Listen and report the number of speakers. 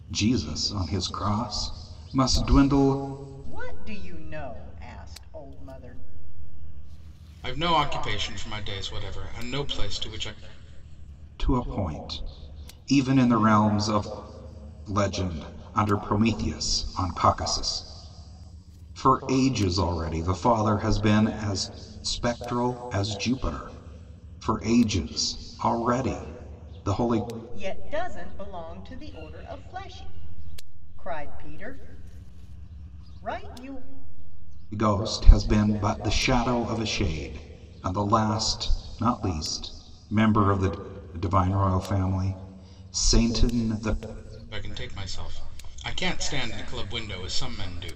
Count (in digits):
3